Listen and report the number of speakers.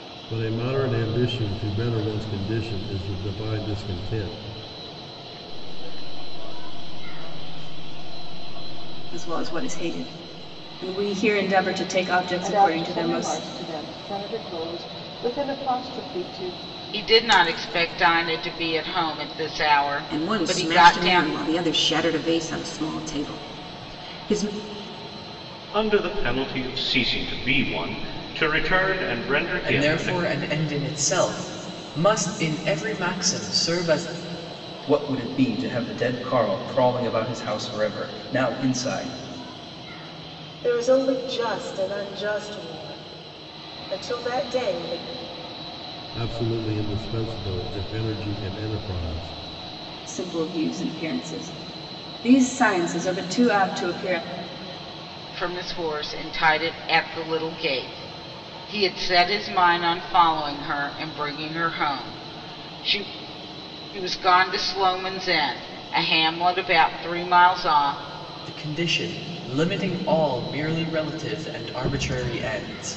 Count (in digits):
10